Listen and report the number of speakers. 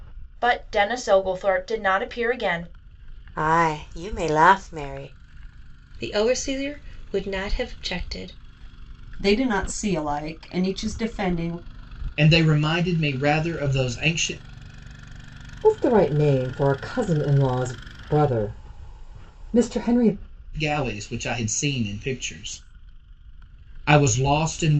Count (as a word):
six